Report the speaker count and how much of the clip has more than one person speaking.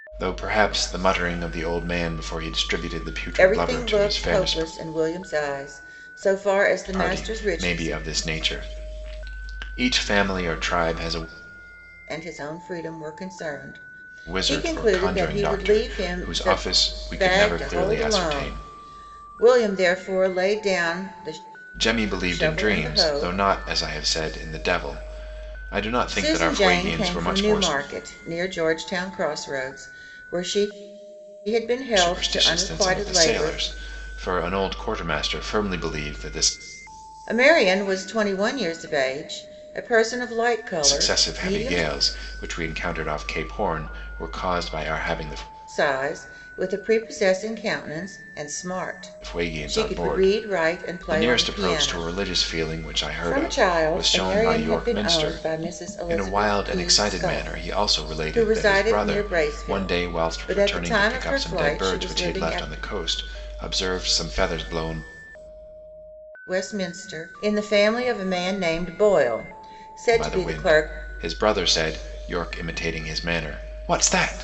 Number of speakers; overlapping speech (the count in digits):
2, about 31%